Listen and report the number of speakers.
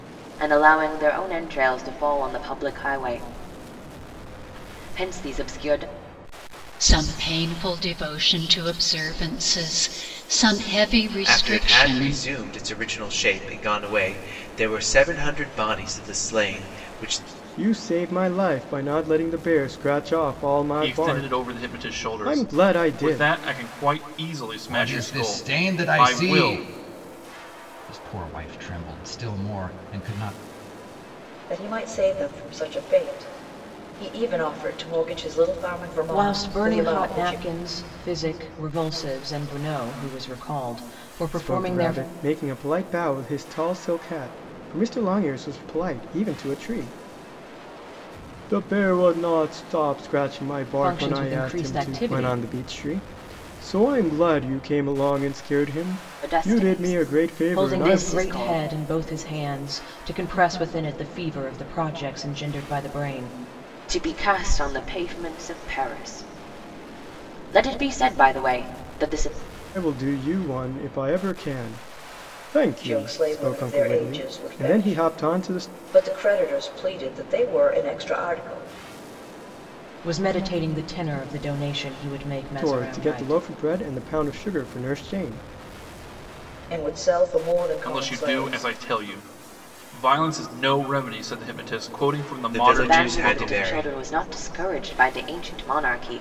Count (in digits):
8